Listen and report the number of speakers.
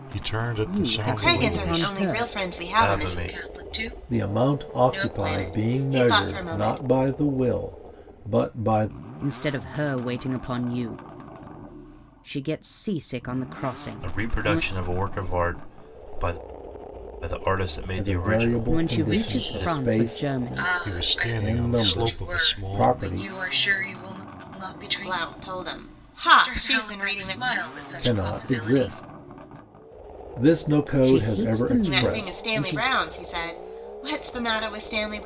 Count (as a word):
six